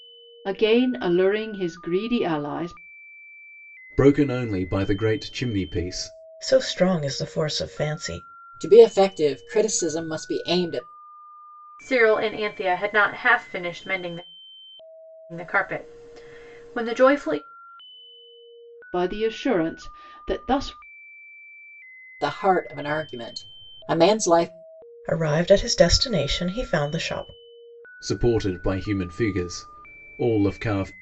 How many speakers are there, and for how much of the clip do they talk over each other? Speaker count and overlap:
5, no overlap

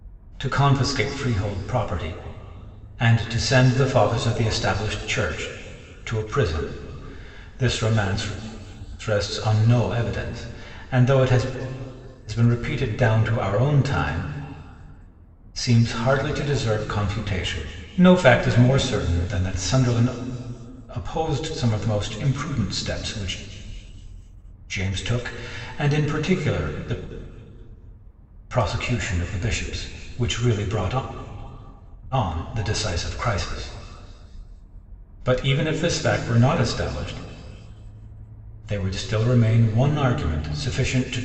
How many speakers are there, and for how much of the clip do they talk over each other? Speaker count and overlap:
1, no overlap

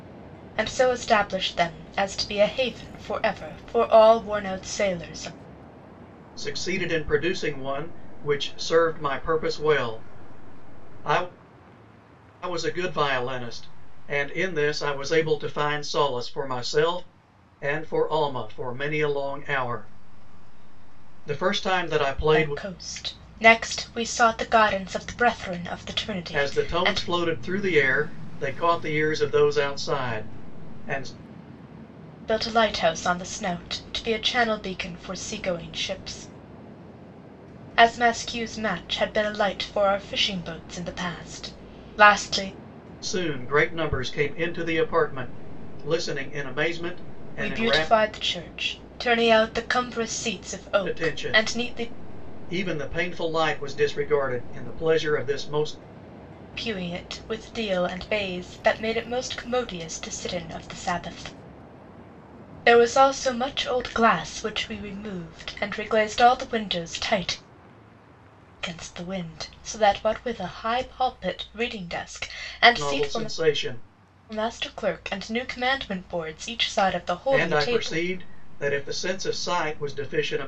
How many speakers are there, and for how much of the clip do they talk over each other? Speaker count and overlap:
2, about 5%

